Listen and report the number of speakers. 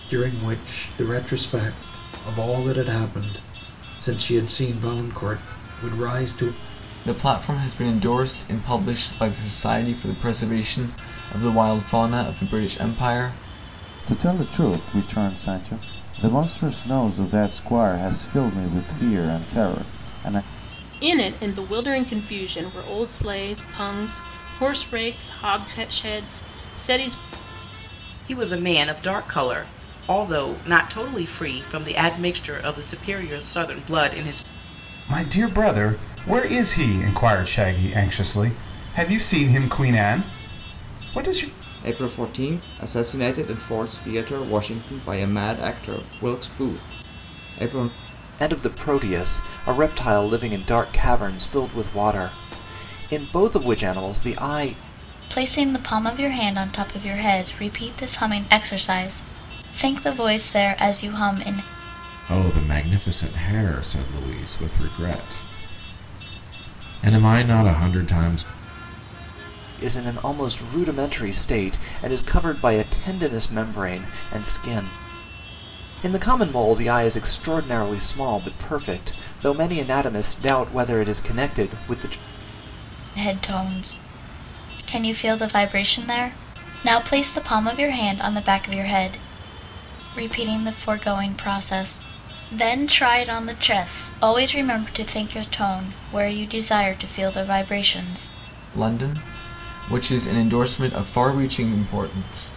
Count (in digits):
10